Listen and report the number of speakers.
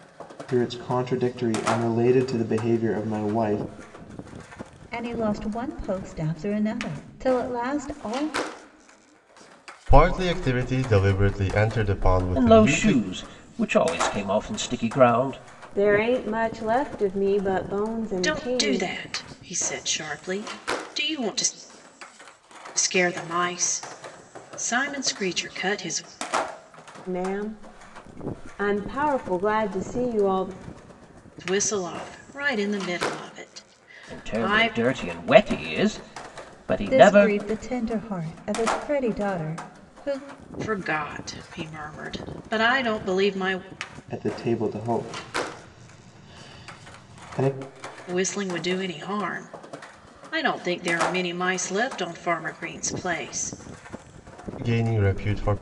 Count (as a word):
six